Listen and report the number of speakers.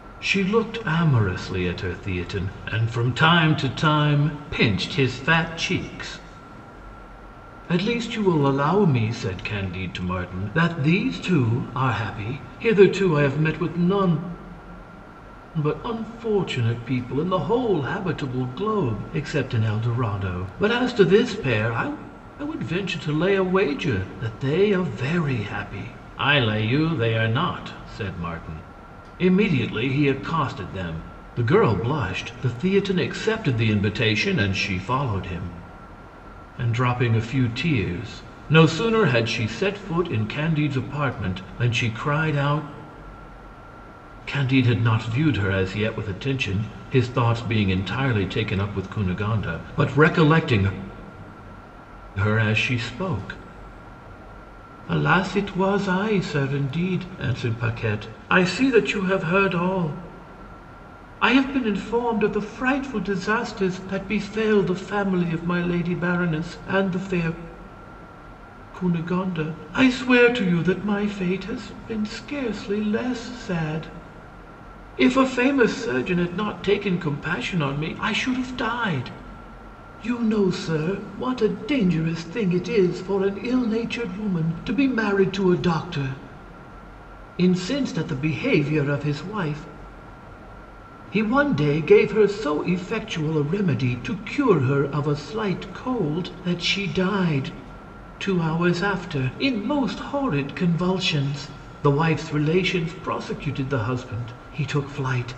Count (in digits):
1